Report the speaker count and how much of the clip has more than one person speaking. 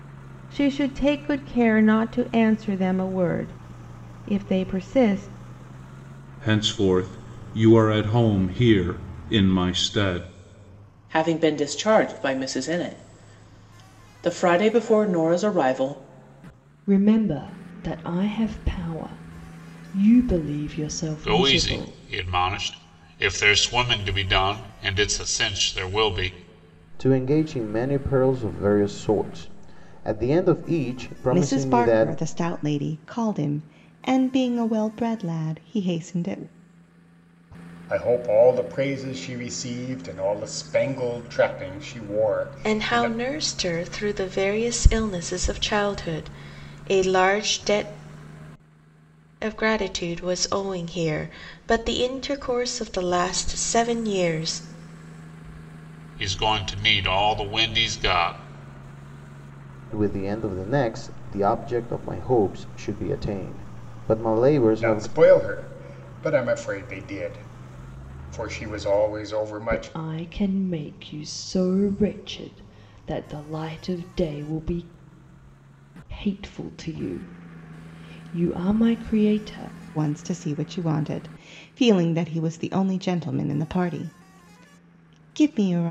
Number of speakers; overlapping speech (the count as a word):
nine, about 3%